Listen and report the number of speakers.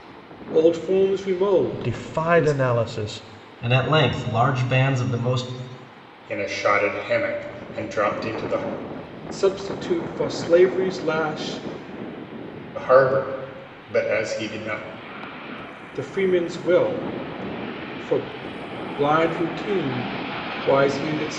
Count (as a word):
four